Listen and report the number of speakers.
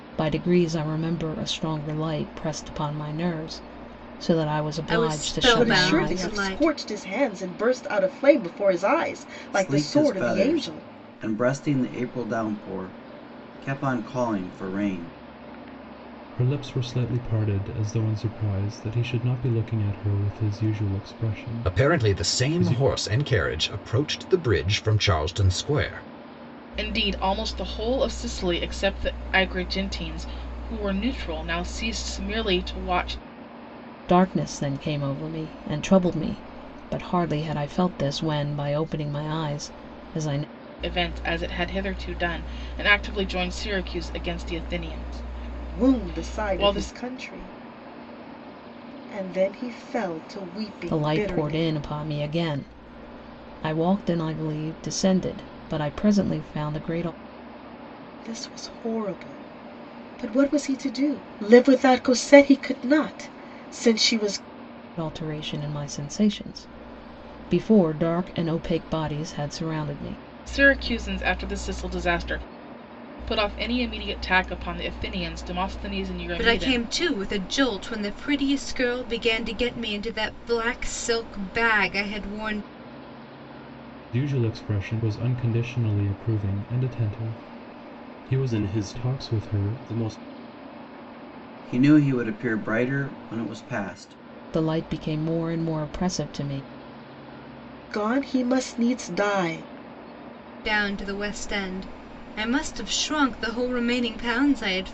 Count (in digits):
7